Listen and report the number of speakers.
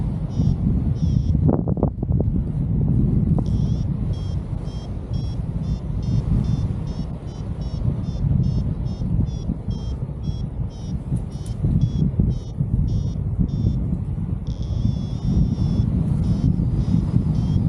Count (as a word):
zero